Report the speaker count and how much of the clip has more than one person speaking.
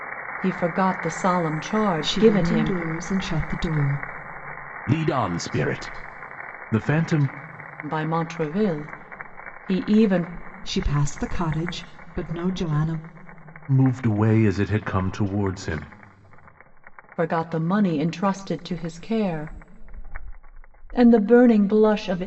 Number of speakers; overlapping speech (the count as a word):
three, about 3%